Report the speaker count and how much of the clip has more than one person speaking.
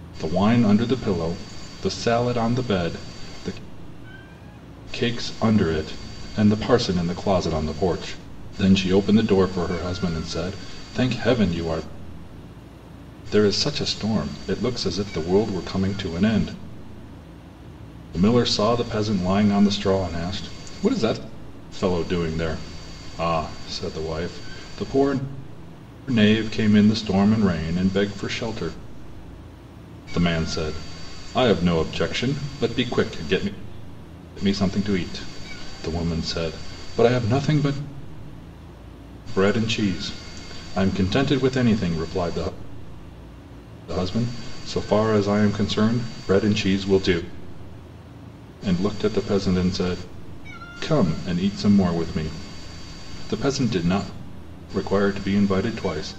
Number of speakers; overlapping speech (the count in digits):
1, no overlap